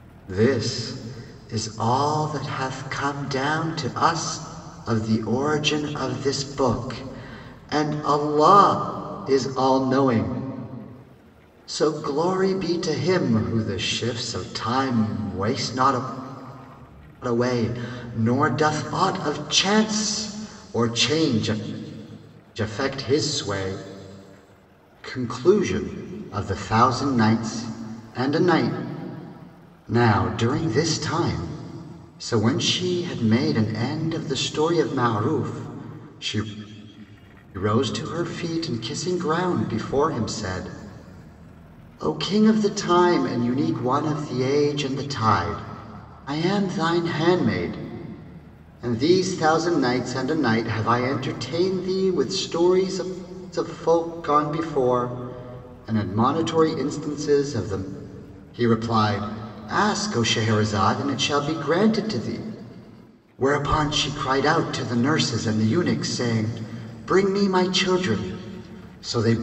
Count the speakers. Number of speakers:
1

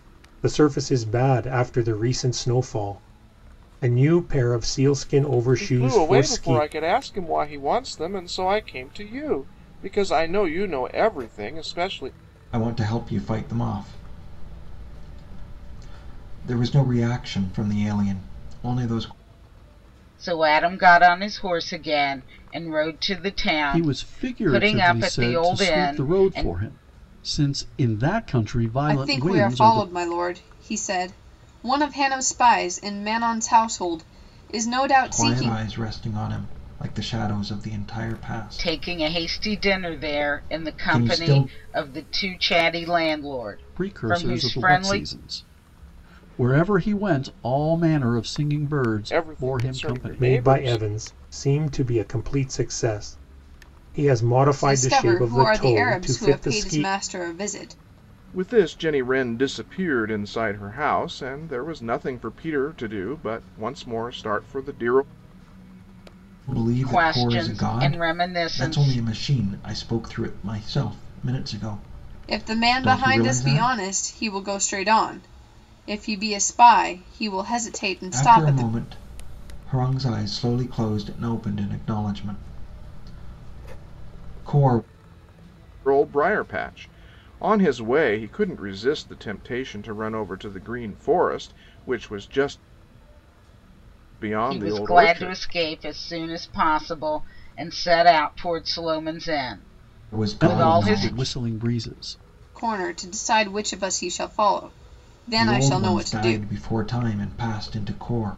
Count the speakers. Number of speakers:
6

